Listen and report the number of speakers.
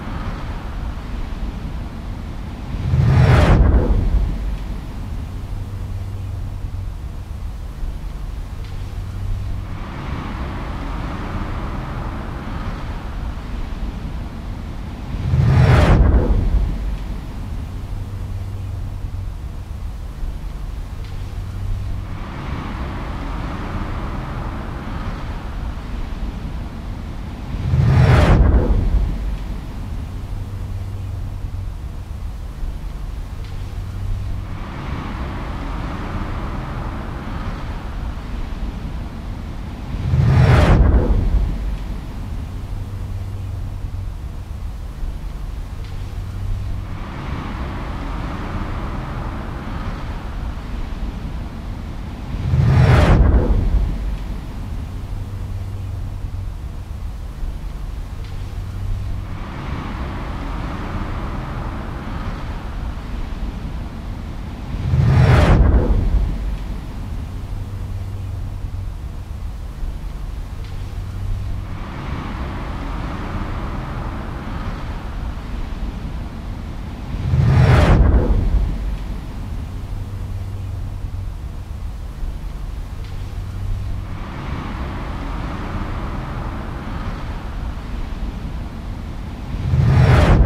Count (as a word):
zero